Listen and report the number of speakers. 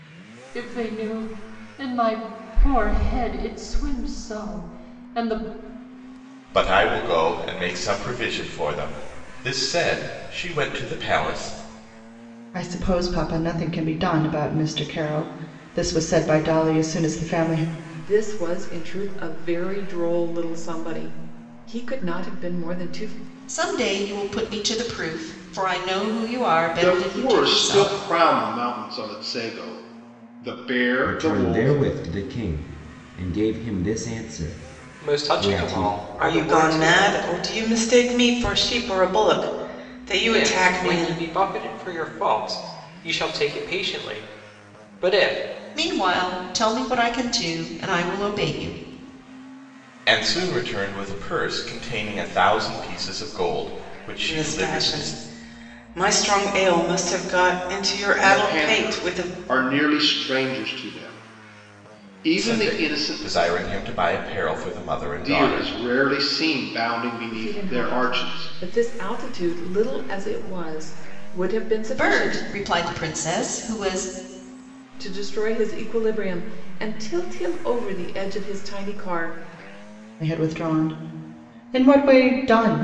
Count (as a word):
nine